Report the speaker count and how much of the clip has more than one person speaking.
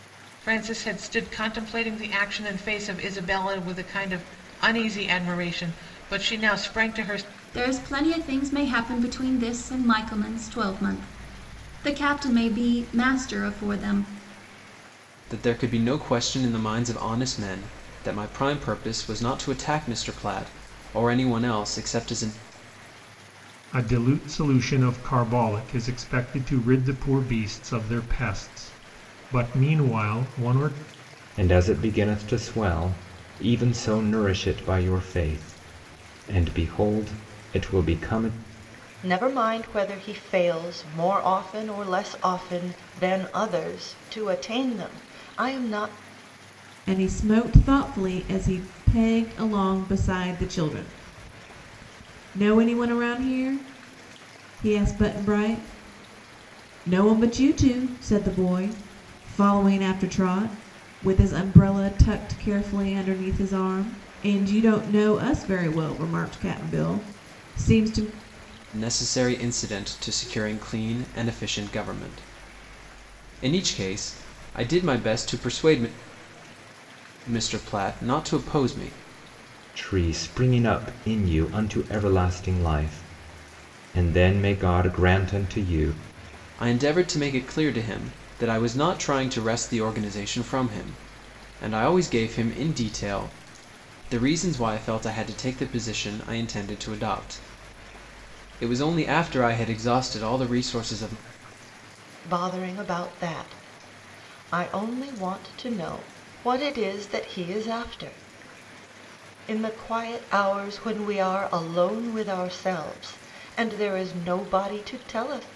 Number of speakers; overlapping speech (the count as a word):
seven, no overlap